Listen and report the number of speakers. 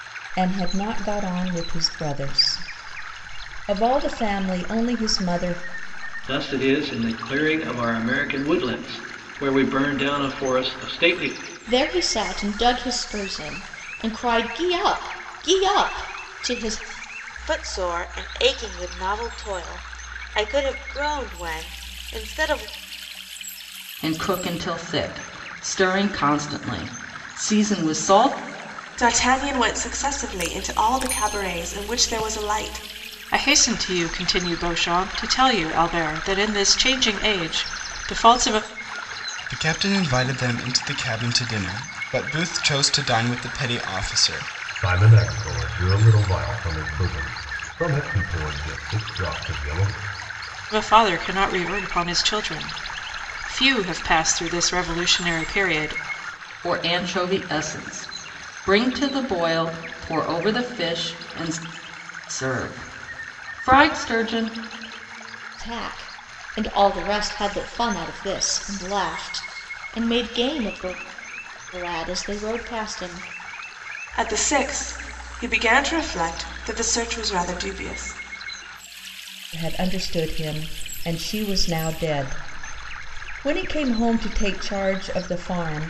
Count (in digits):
9